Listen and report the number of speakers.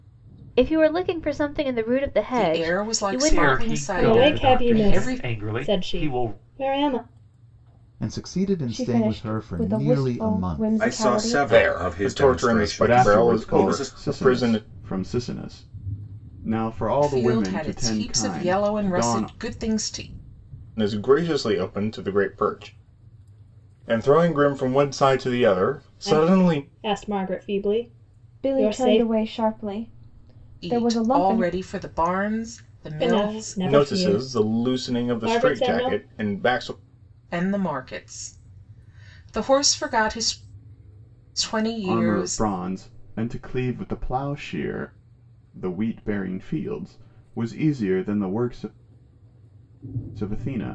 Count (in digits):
9